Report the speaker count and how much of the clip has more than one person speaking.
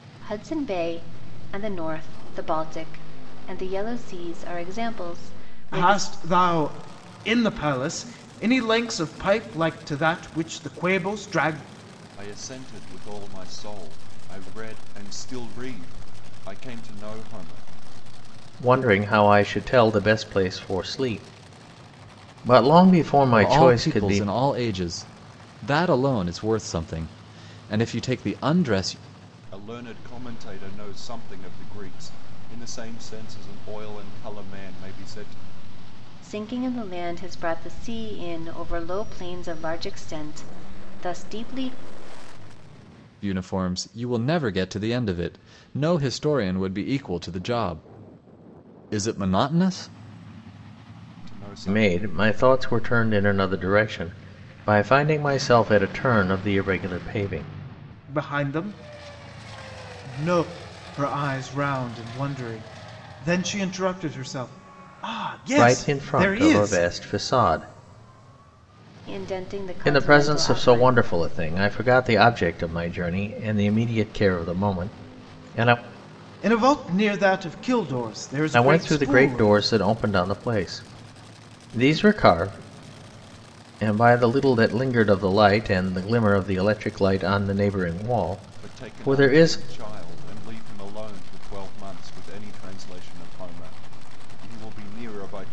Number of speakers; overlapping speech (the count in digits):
5, about 7%